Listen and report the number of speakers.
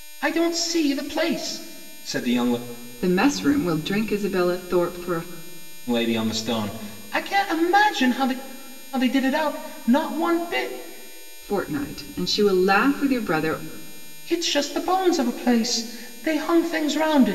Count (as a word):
two